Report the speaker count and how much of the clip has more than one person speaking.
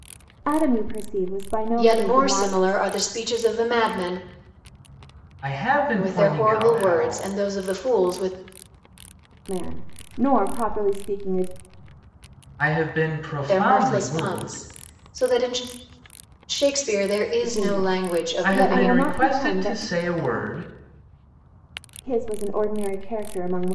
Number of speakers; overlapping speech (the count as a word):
three, about 25%